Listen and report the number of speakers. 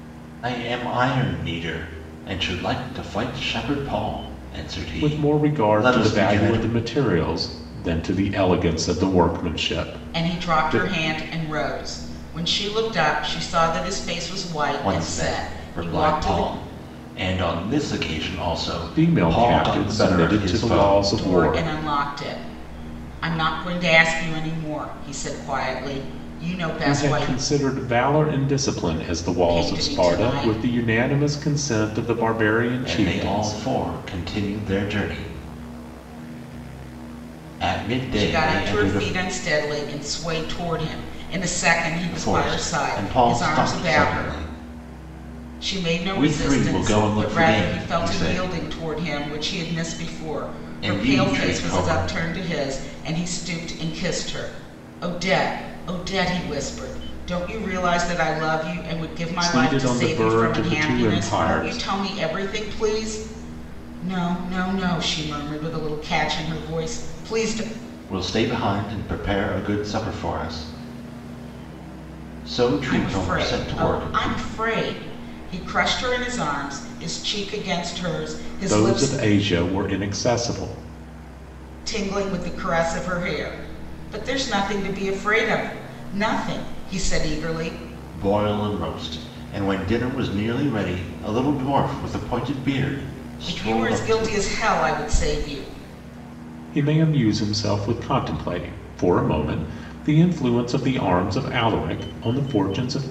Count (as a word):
three